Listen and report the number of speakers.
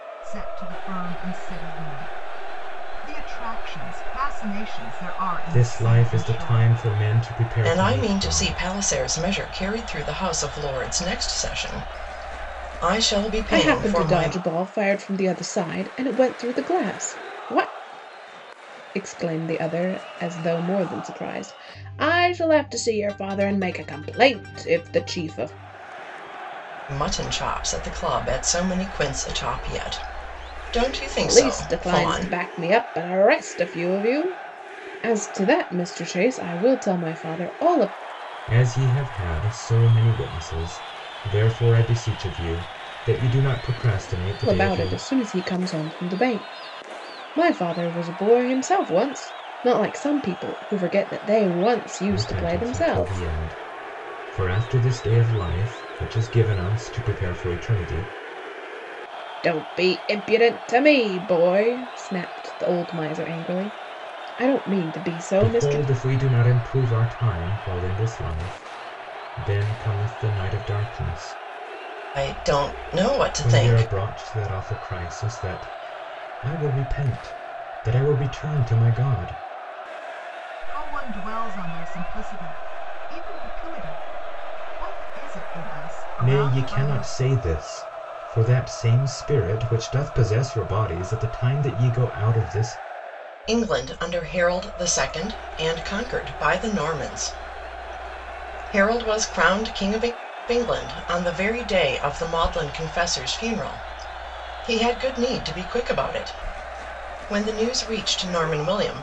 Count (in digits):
4